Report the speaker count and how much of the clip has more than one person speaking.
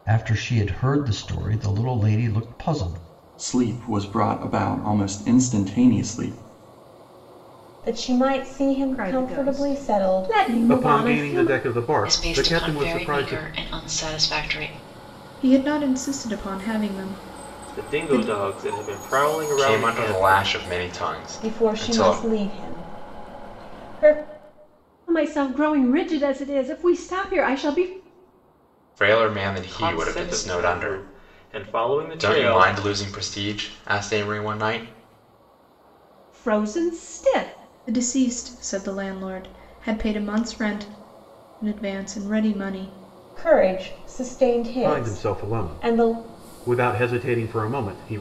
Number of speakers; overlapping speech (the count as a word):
nine, about 20%